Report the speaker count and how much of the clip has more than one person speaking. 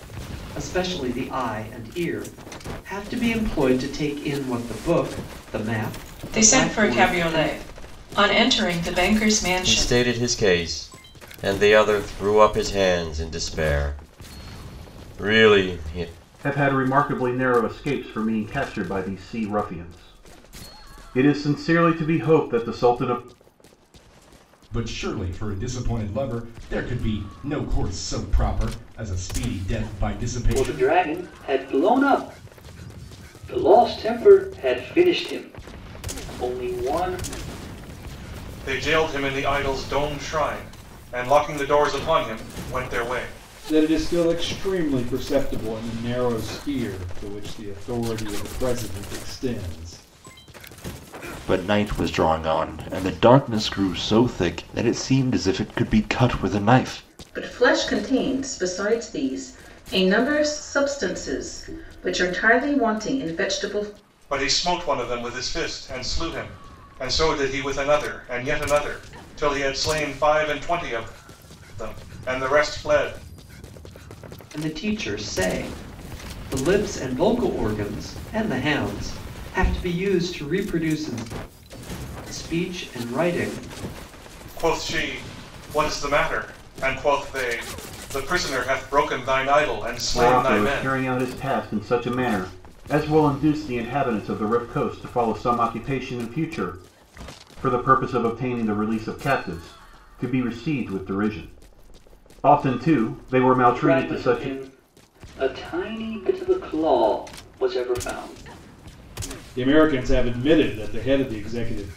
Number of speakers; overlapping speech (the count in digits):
10, about 3%